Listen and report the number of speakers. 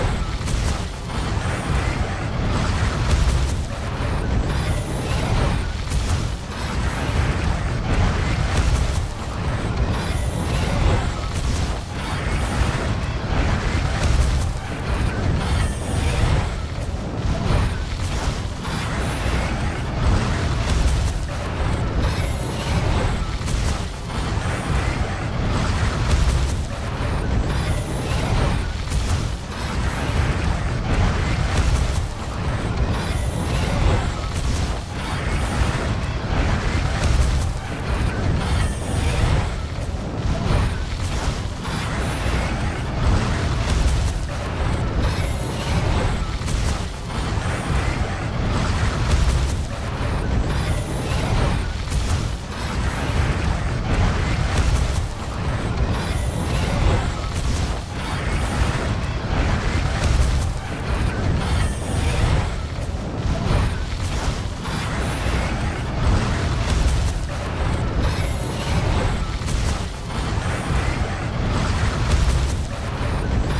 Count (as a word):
zero